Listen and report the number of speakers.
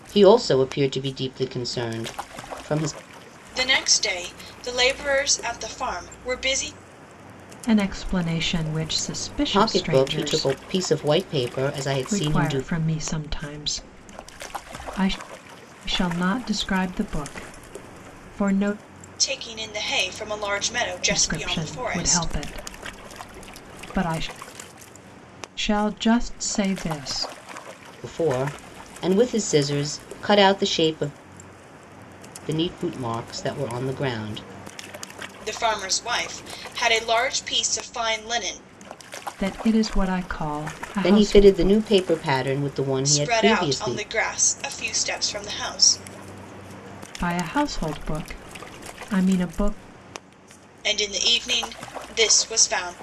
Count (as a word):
three